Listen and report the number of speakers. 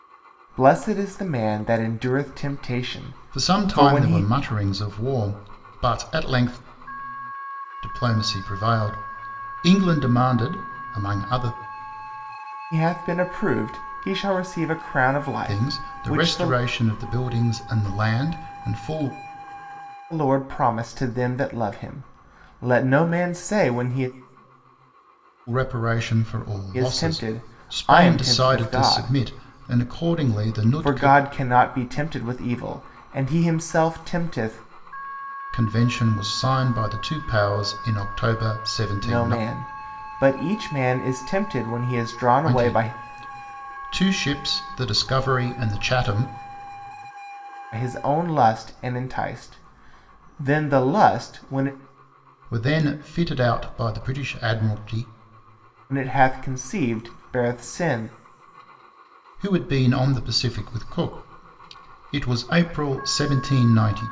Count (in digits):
2